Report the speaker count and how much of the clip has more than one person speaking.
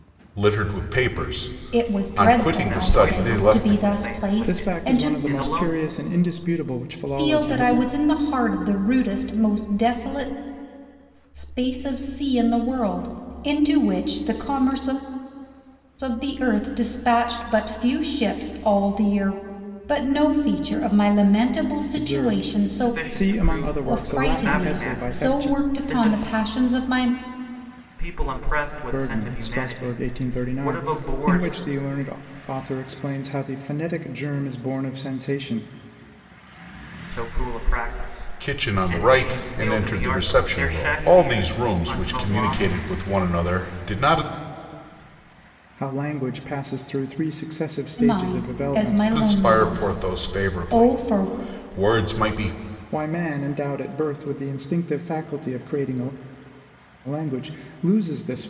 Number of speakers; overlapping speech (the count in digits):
4, about 33%